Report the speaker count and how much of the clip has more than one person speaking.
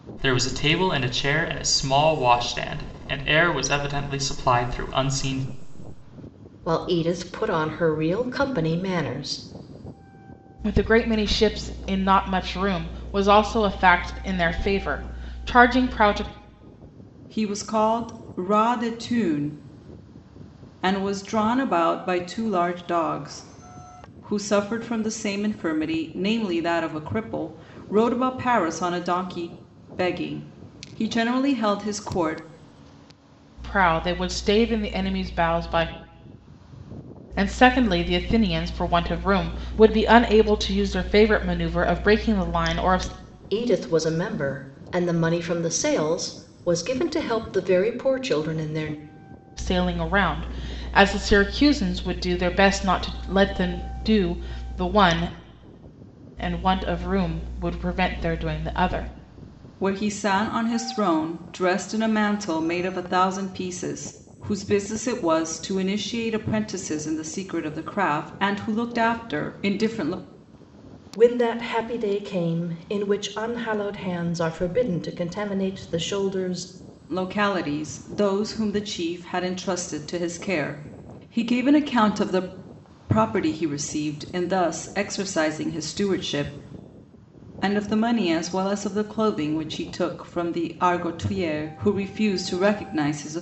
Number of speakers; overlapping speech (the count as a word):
four, no overlap